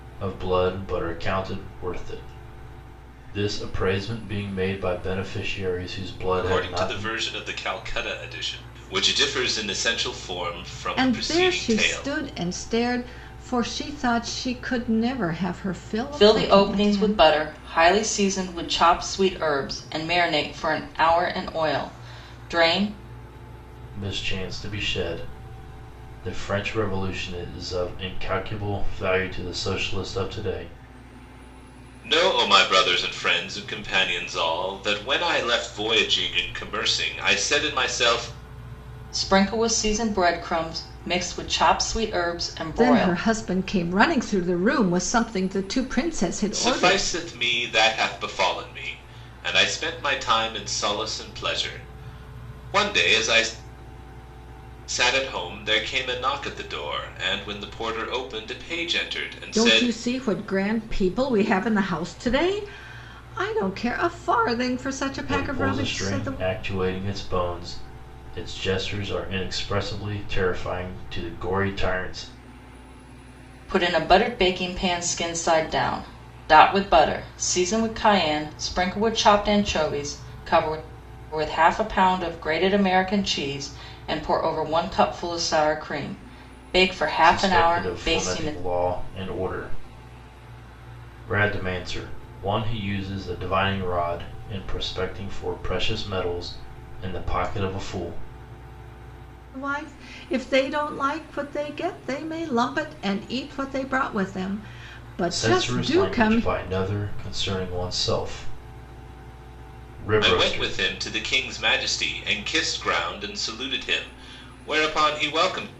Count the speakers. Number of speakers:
4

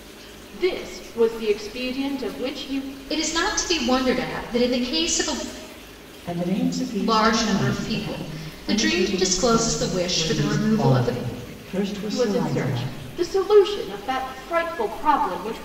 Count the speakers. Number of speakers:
3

